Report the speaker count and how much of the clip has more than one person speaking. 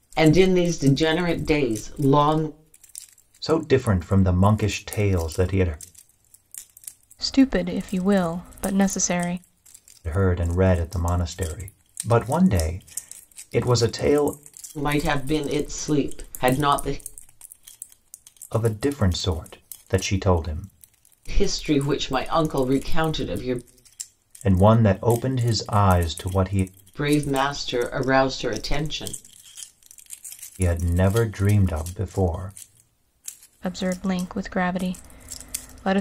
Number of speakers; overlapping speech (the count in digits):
3, no overlap